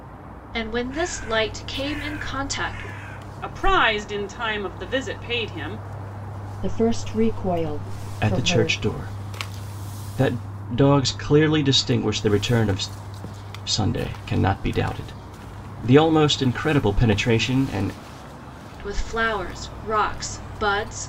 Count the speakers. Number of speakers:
4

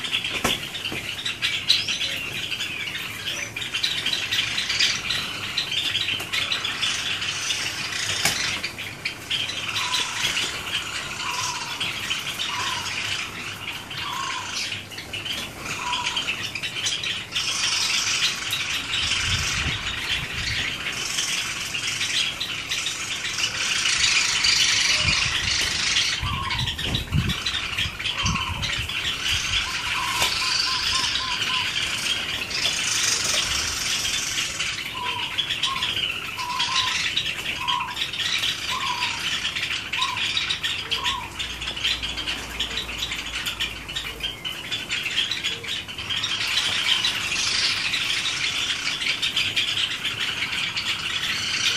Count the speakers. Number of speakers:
0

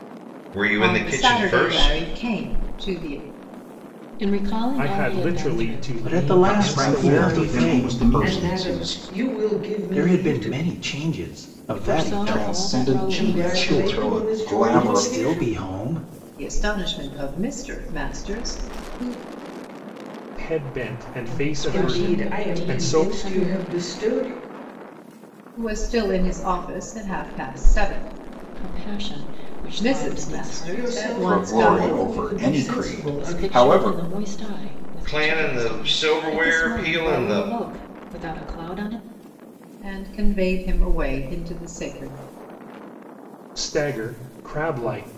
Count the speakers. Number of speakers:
8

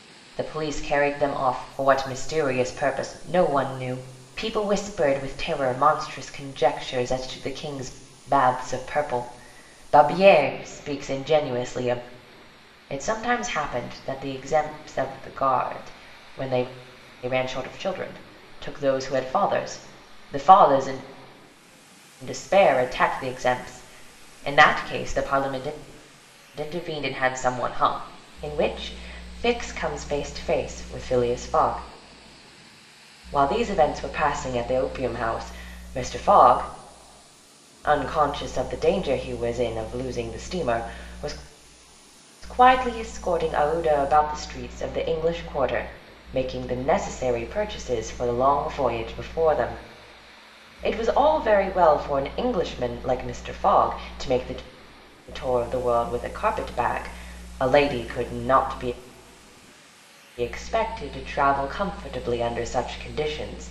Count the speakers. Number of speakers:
1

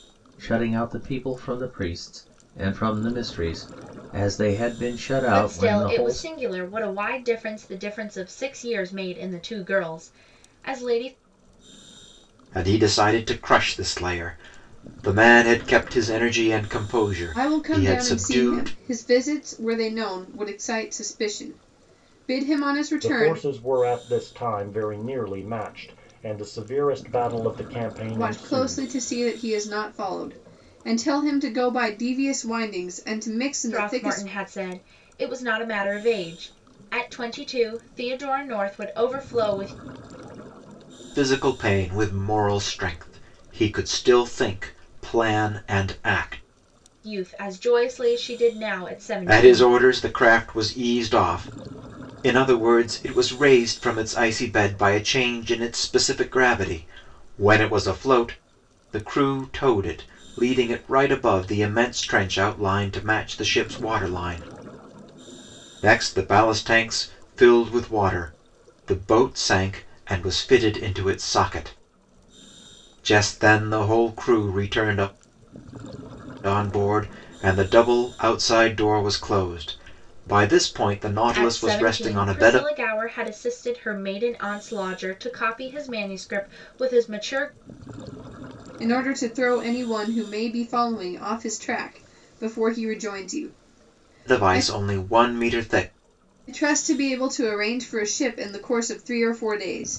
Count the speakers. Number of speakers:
5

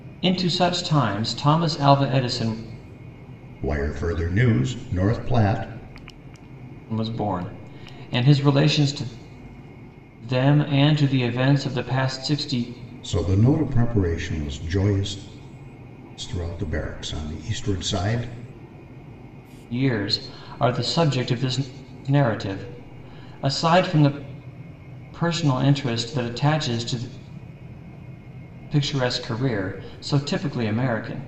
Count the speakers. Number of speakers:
2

